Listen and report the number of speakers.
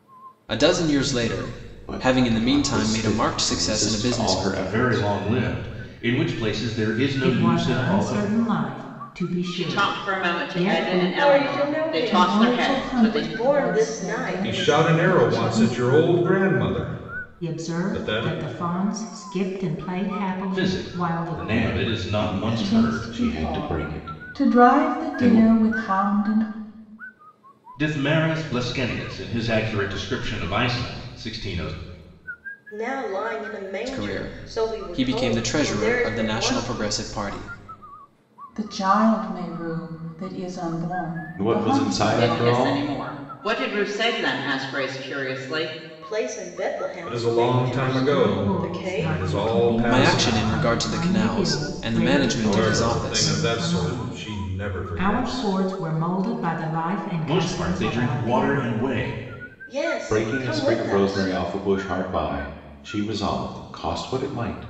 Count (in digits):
8